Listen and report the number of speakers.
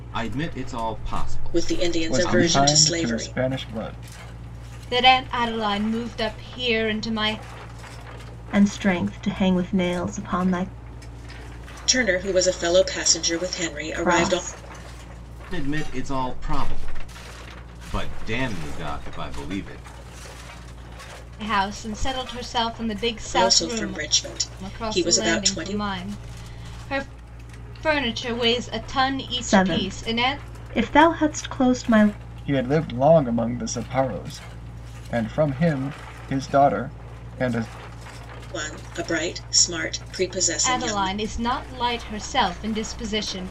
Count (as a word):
five